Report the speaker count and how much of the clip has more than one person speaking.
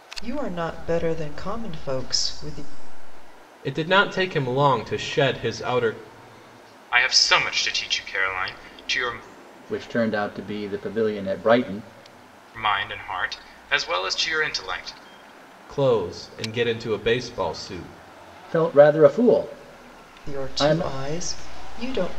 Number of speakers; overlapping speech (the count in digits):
4, about 3%